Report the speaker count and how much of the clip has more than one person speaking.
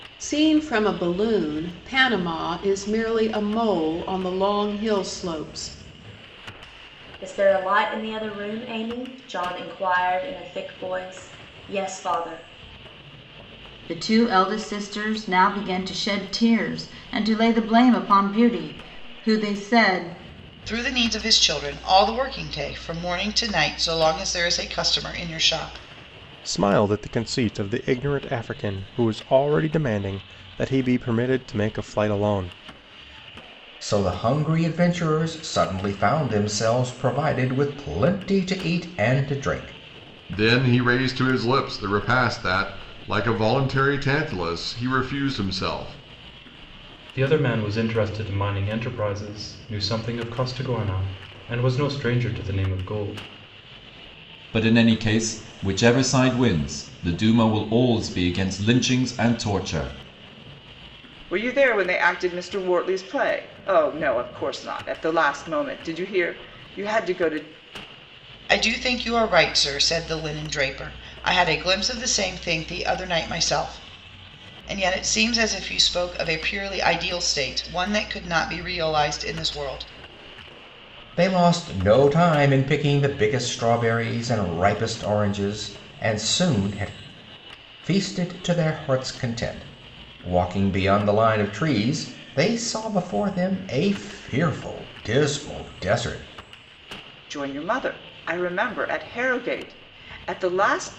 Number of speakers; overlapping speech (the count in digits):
10, no overlap